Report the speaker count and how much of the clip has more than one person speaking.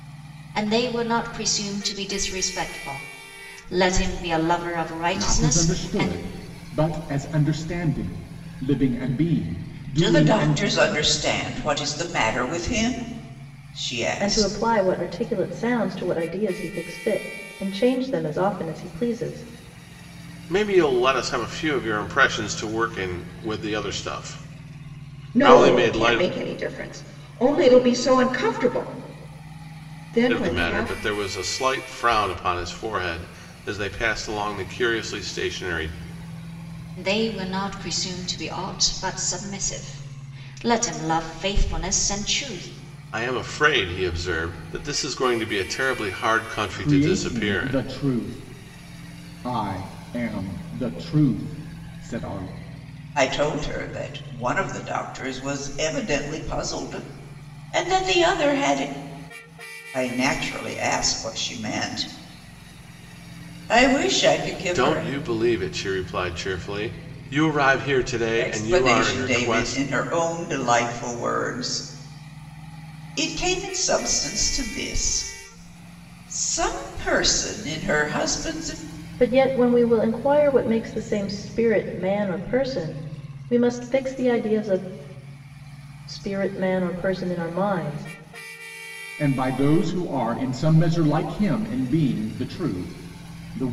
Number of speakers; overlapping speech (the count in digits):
6, about 7%